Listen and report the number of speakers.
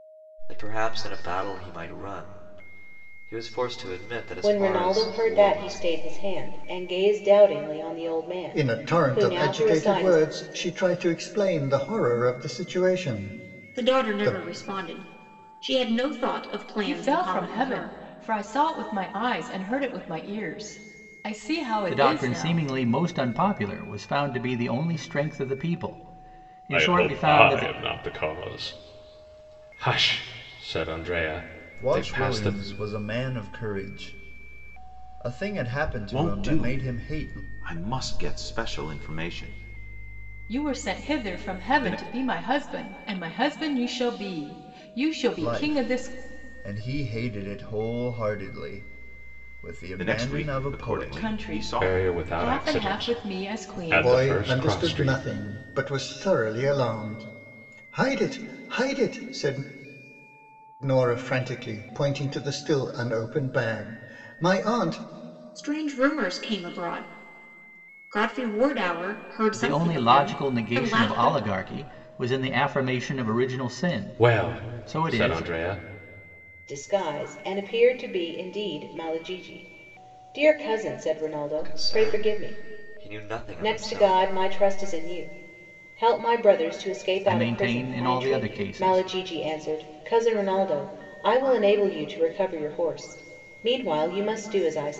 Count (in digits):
9